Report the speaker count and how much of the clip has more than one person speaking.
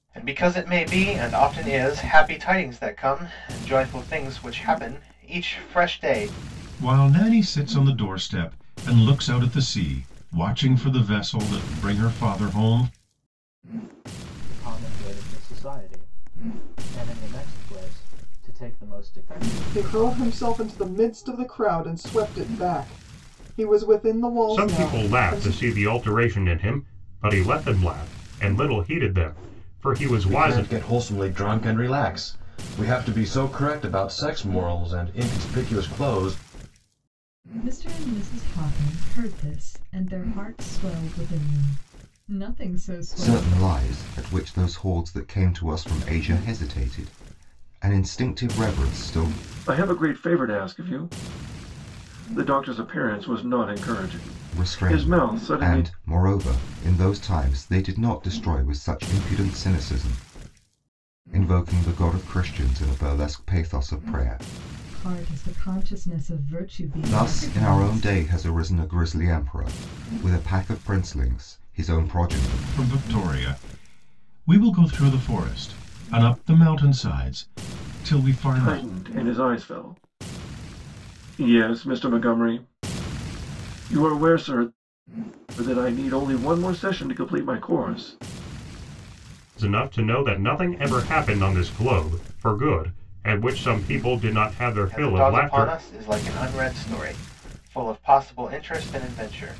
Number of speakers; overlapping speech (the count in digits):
9, about 7%